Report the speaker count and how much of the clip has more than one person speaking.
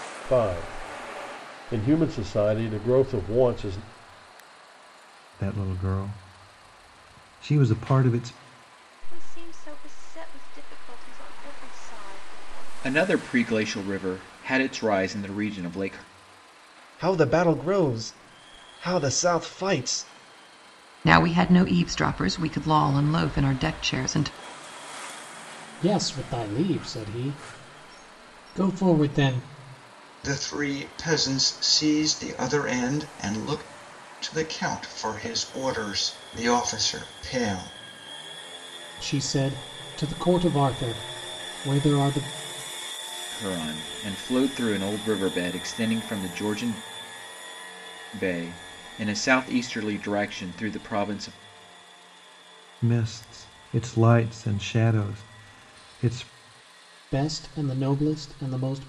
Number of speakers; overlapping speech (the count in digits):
8, no overlap